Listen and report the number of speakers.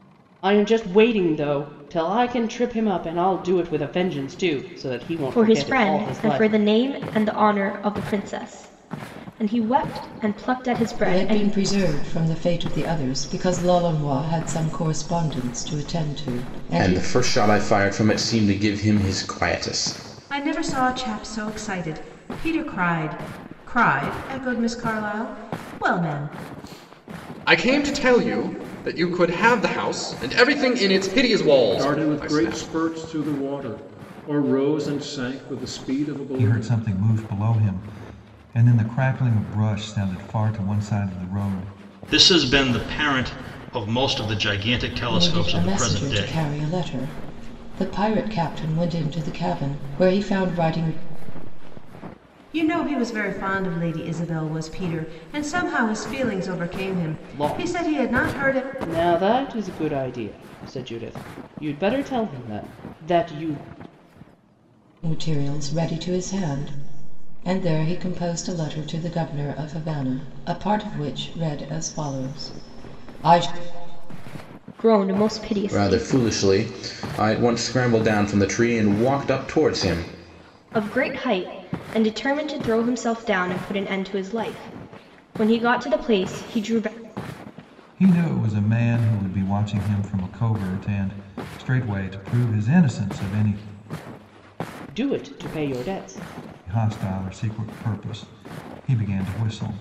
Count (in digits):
9